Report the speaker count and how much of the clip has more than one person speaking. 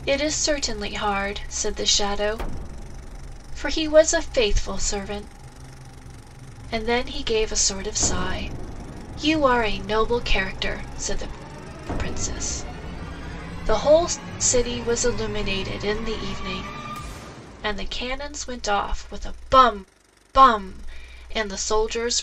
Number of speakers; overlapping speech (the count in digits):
1, no overlap